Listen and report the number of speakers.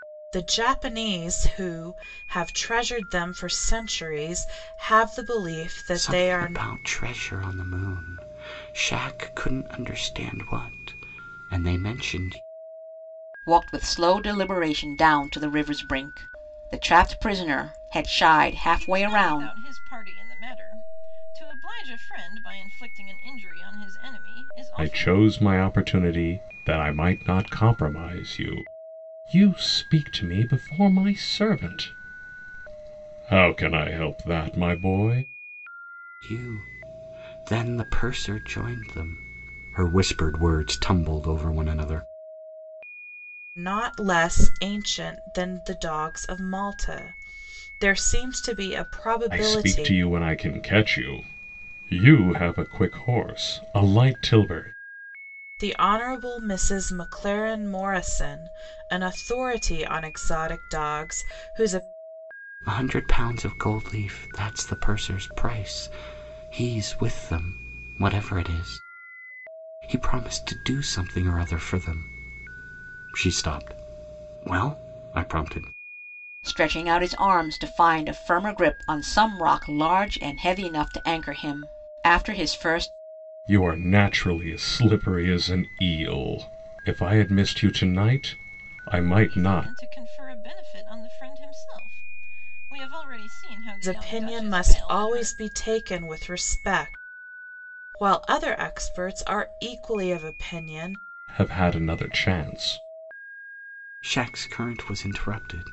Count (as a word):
five